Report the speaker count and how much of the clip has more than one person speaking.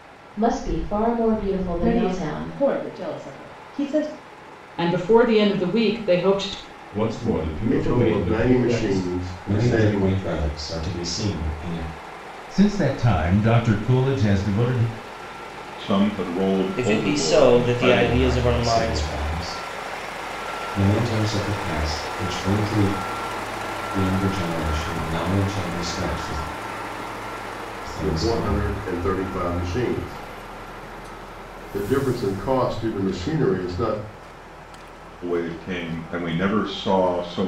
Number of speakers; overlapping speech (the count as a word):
nine, about 16%